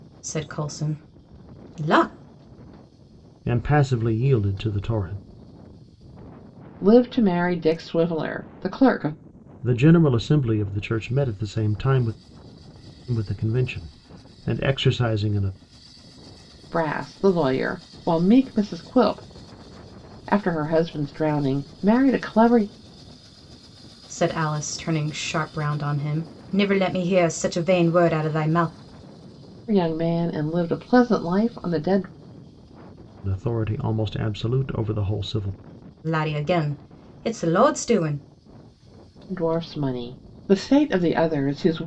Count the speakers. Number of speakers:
3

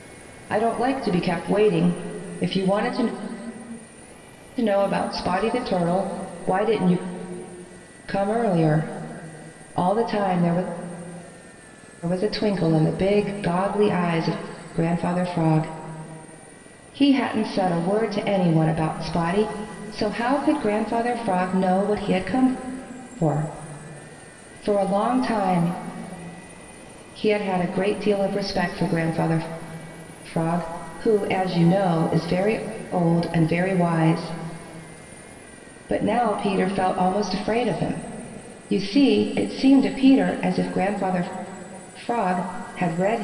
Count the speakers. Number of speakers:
1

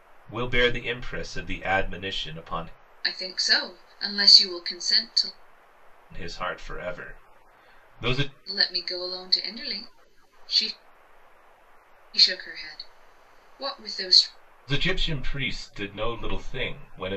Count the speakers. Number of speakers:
2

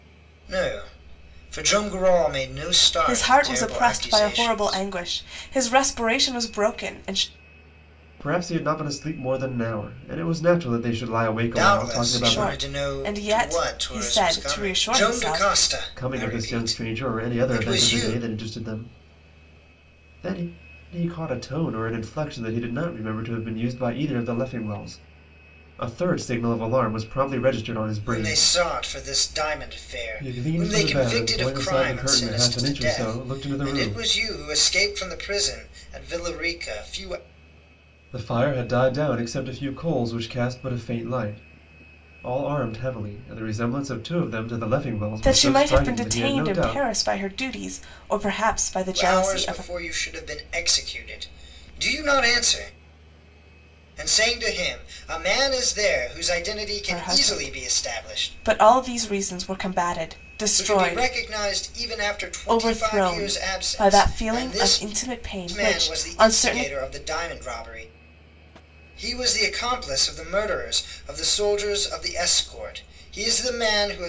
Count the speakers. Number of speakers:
3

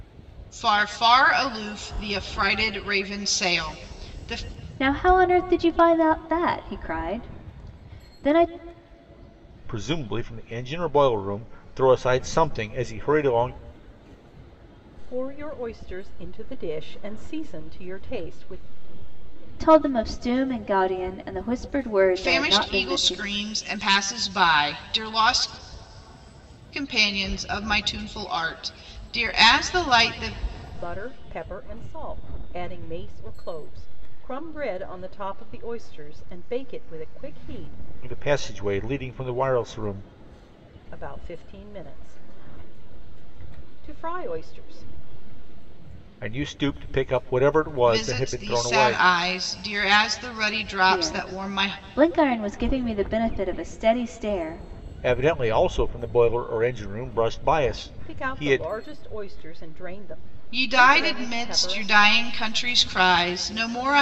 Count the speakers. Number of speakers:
4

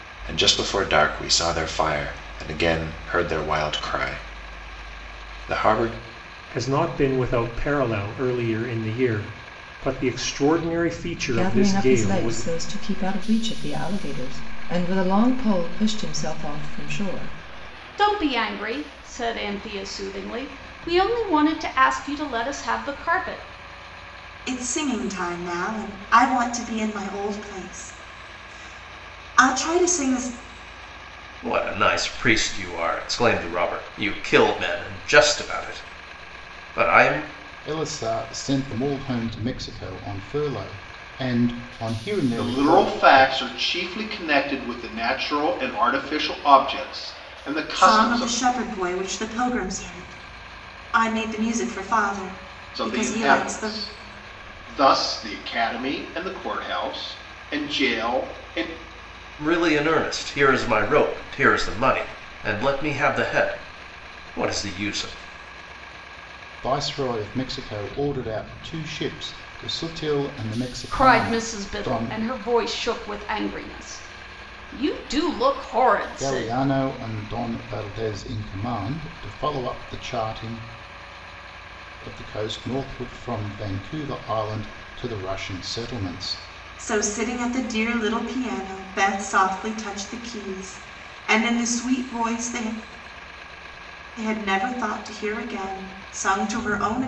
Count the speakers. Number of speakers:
8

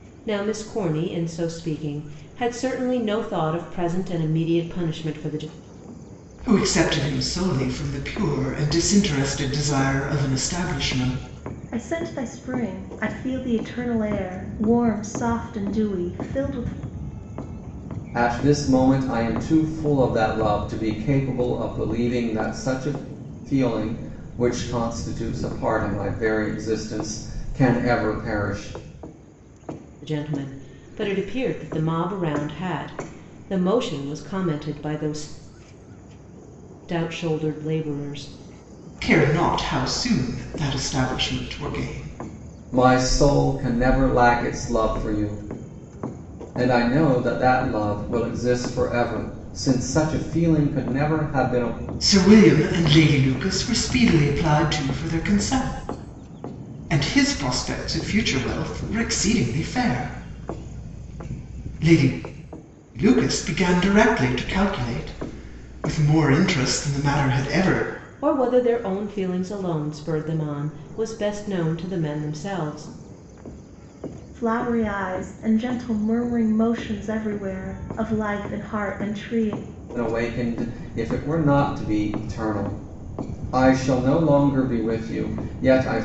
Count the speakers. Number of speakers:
4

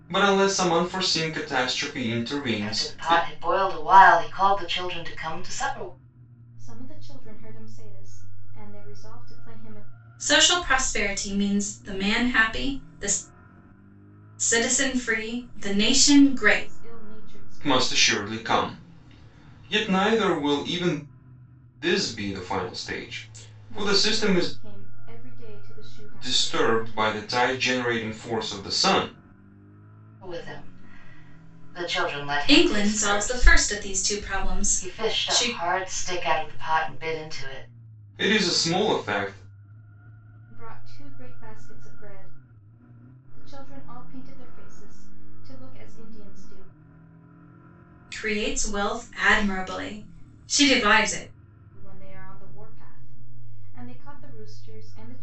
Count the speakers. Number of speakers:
4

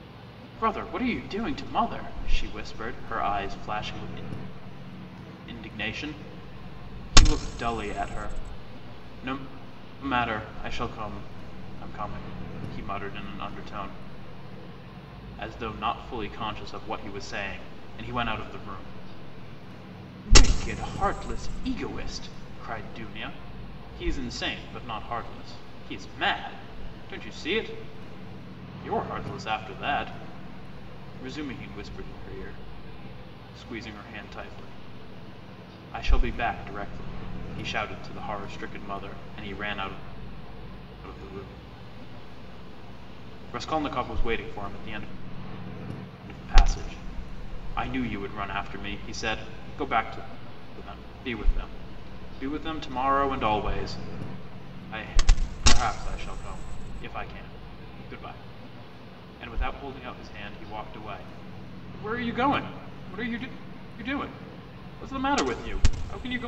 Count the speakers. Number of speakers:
1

